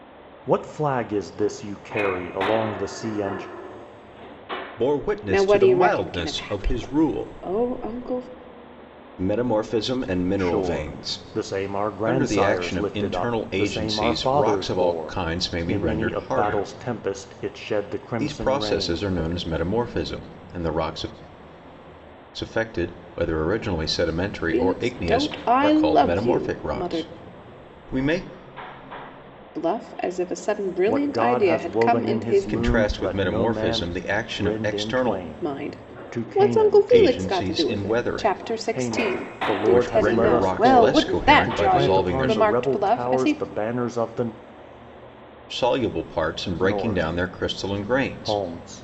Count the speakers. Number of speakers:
three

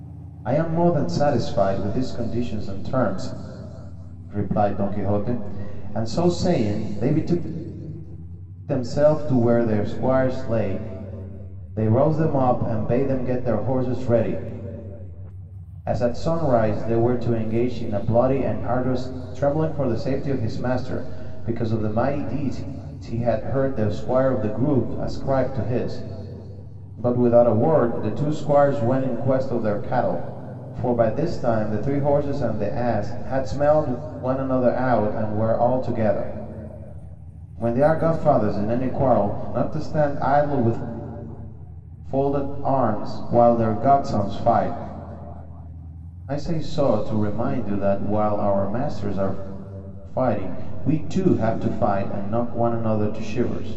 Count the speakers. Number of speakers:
one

